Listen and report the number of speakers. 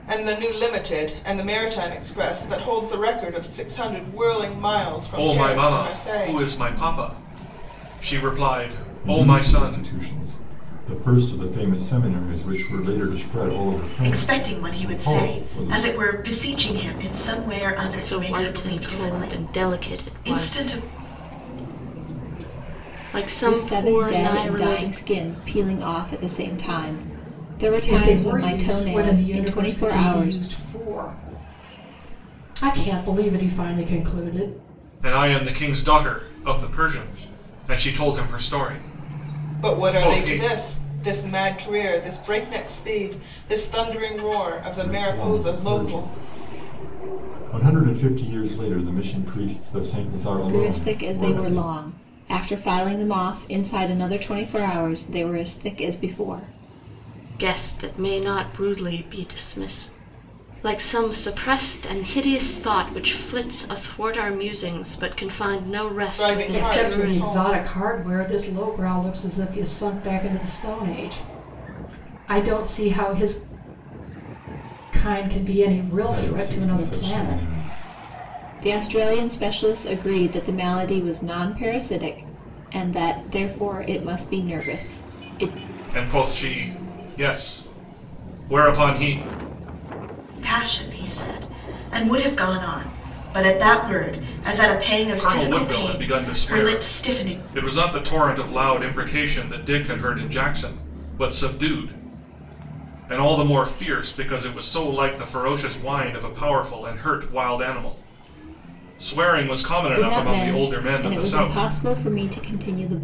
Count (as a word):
seven